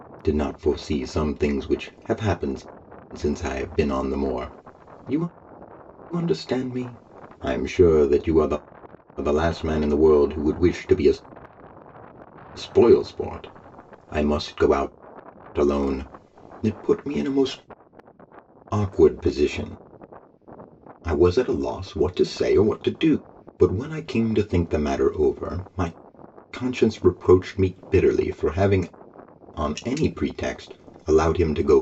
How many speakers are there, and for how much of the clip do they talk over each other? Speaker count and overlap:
one, no overlap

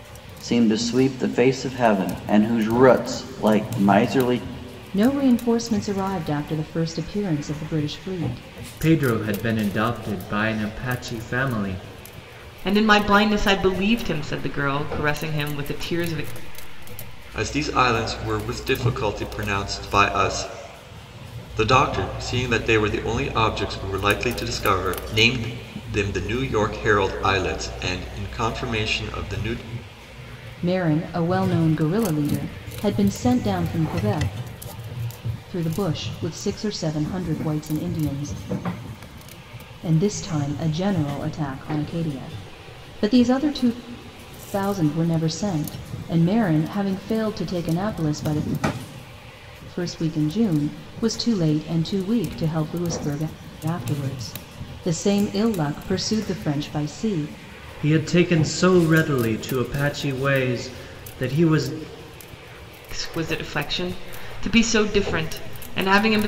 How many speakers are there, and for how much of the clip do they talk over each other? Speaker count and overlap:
five, no overlap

